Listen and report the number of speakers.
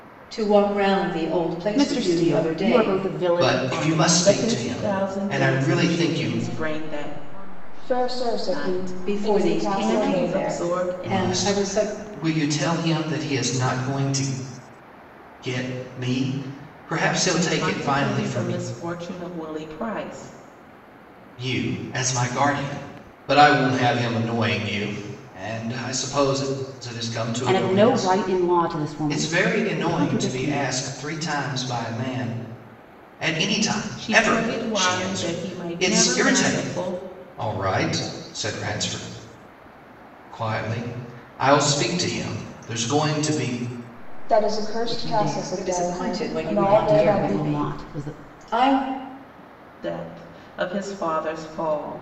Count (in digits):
6